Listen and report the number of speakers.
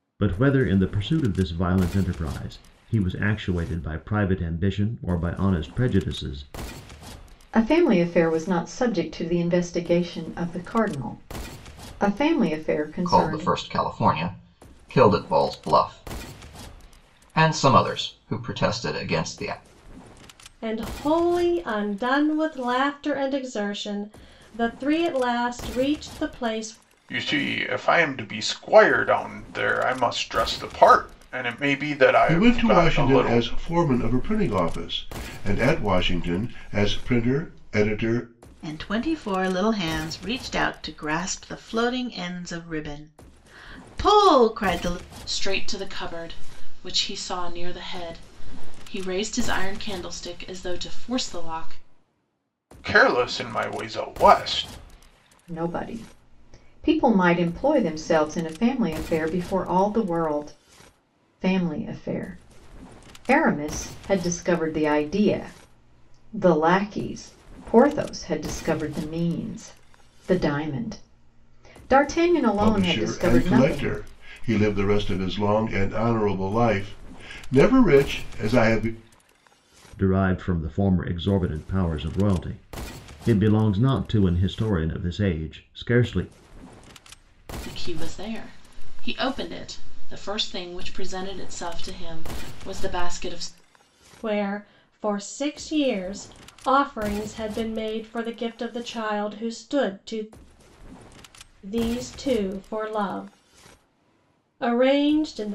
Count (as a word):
eight